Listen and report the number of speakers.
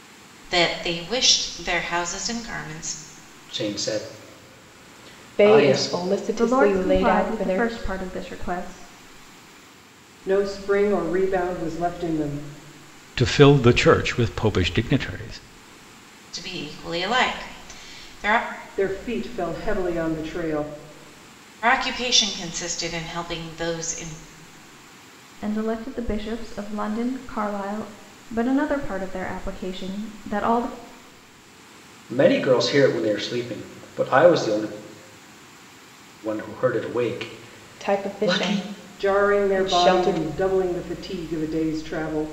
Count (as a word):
six